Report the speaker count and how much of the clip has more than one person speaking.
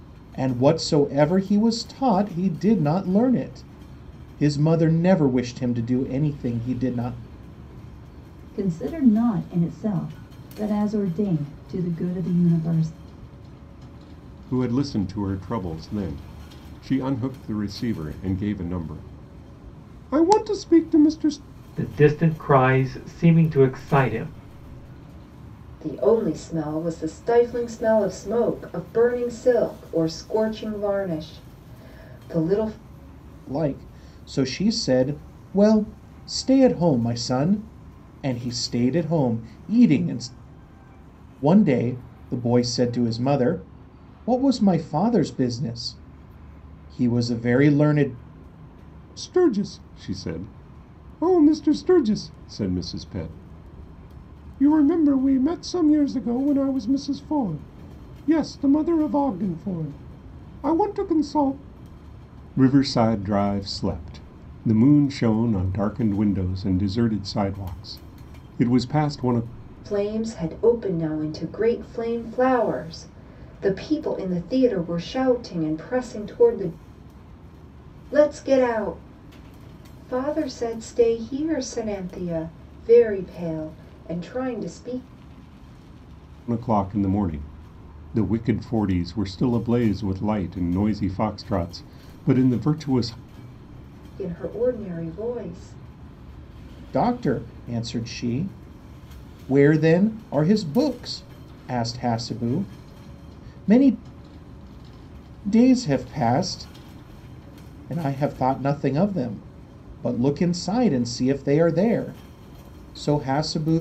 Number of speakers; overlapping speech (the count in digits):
5, no overlap